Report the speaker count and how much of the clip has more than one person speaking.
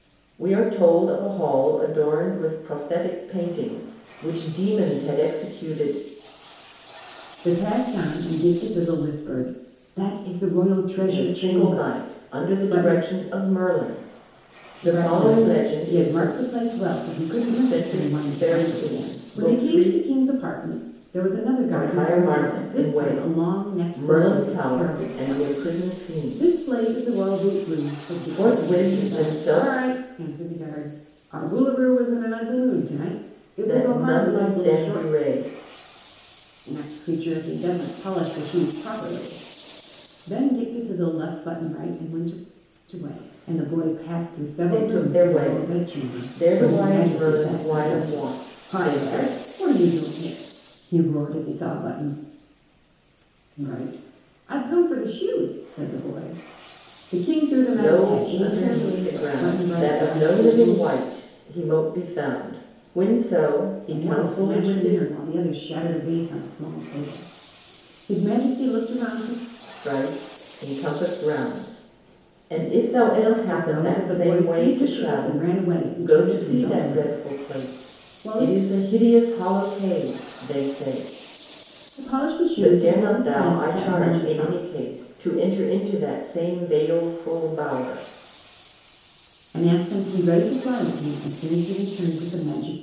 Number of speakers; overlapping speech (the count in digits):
2, about 33%